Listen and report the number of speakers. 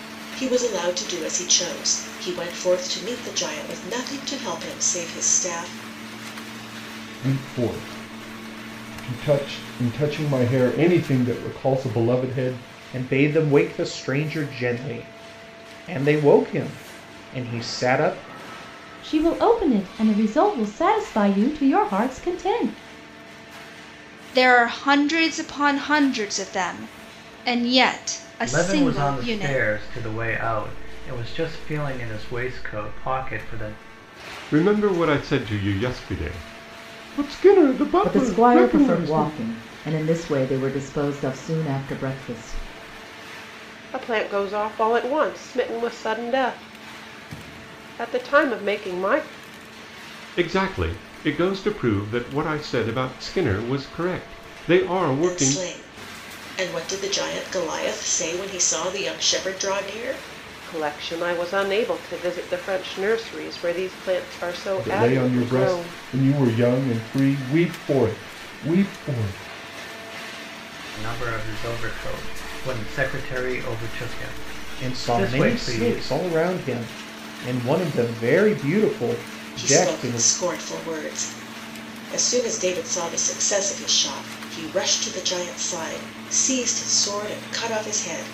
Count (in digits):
9